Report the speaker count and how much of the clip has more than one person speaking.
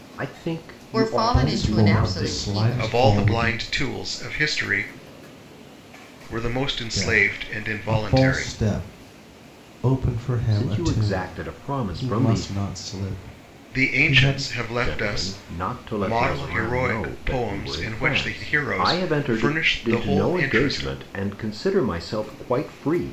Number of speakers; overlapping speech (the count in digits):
4, about 54%